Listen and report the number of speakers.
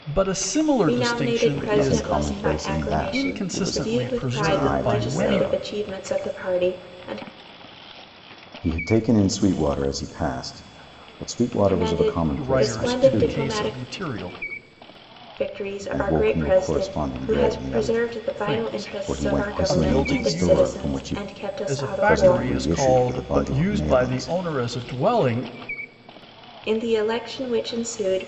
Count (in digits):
3